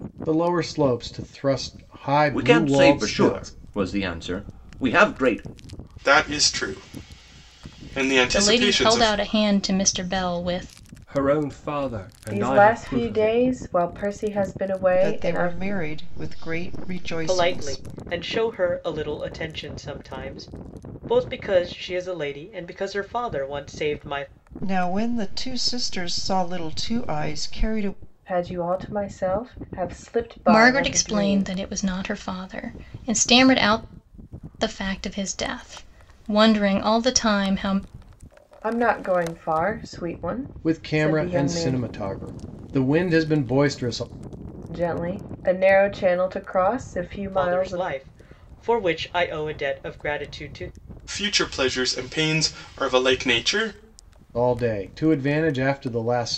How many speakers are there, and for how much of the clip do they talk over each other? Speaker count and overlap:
eight, about 14%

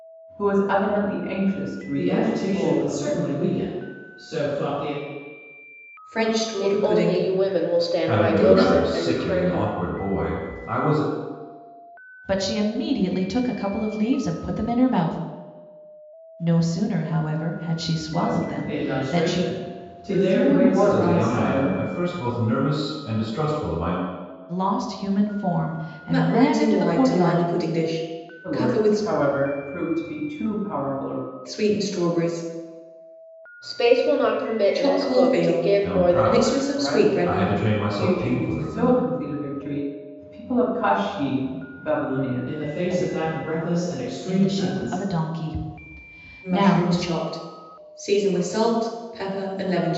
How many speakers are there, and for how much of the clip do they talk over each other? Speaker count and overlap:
six, about 33%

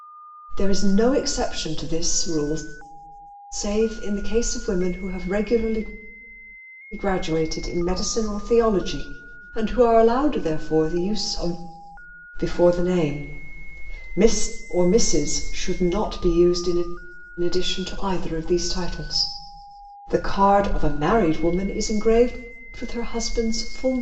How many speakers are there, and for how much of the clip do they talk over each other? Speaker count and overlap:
one, no overlap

